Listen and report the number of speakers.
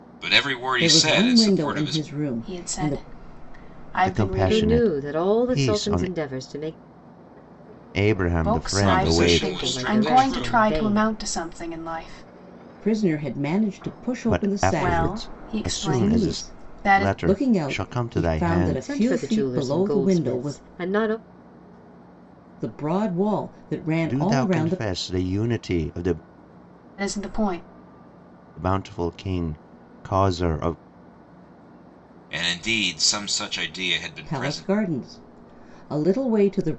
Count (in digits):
5